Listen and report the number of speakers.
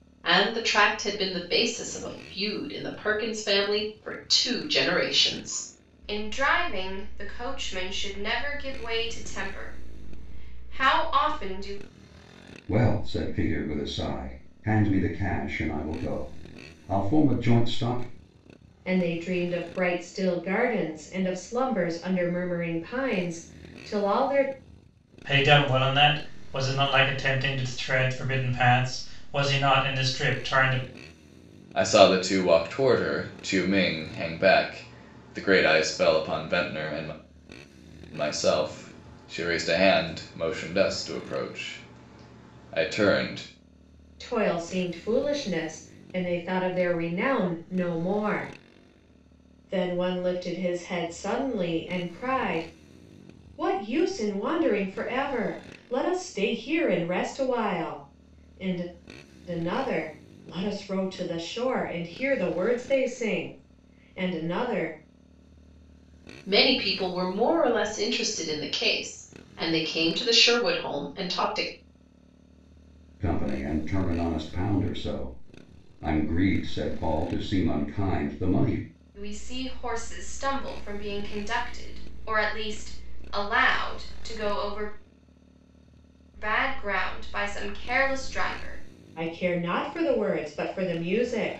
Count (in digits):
6